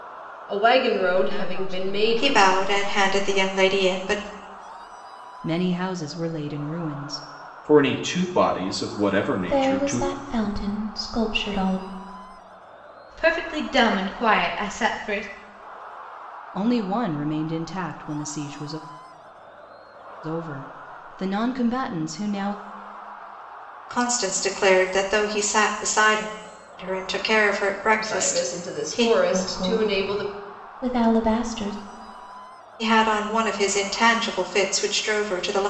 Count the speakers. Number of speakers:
7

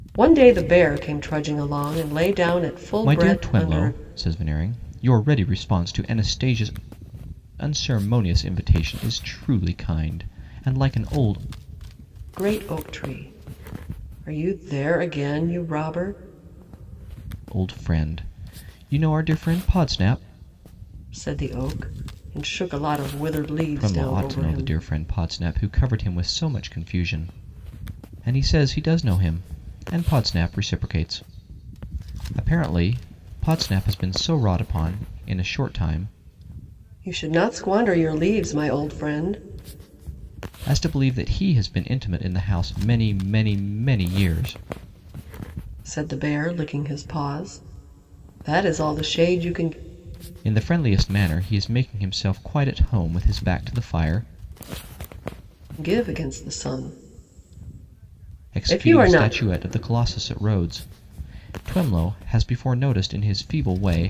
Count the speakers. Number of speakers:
2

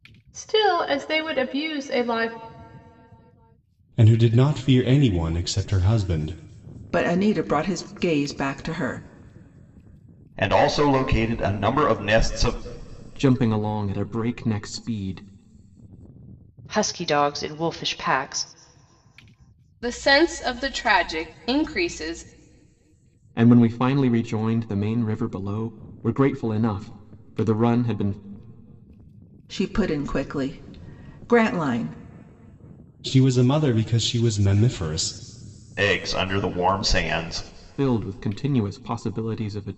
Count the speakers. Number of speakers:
7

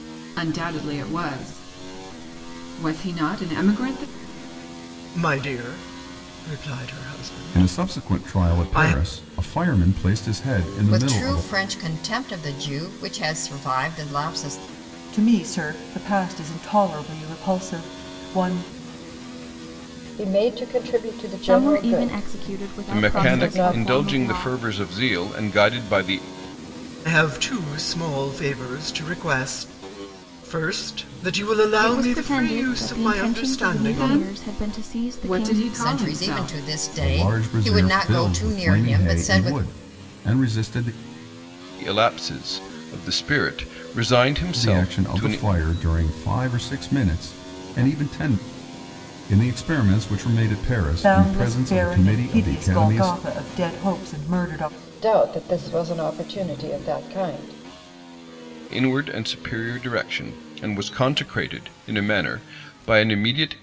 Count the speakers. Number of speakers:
8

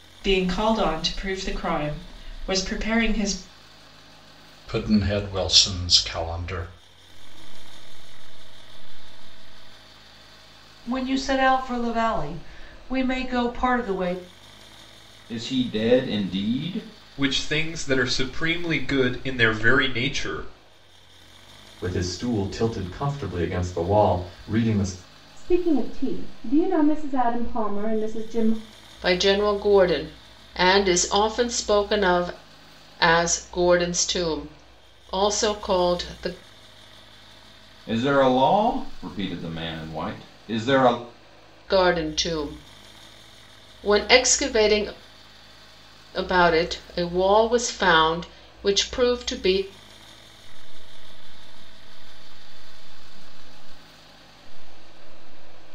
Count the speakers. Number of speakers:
9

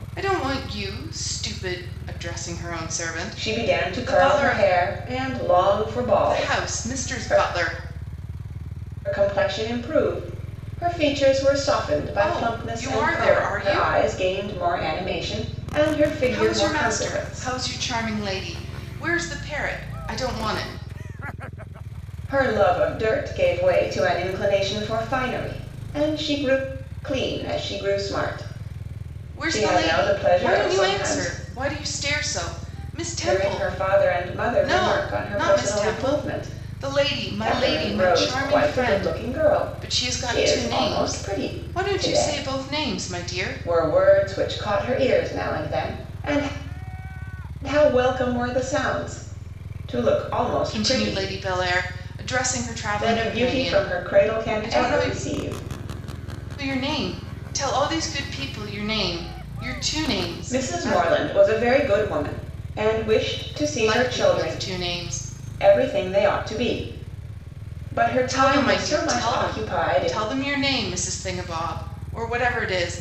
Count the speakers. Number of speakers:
2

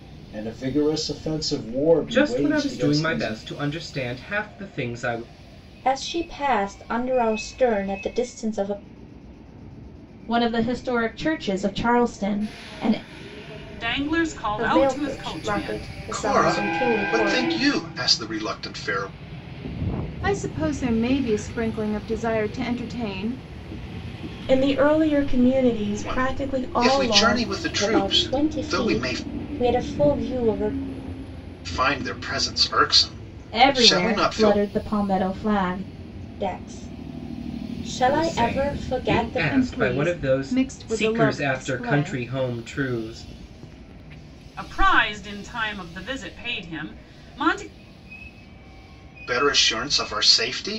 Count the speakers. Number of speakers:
9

